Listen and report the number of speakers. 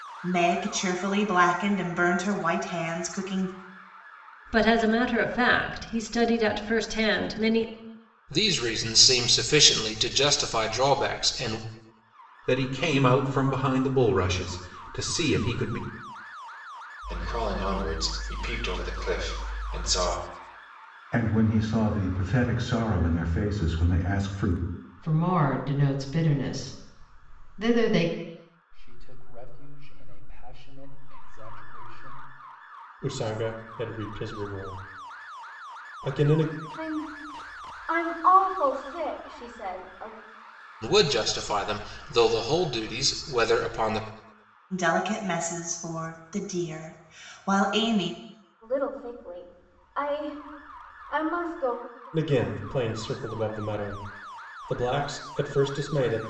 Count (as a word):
ten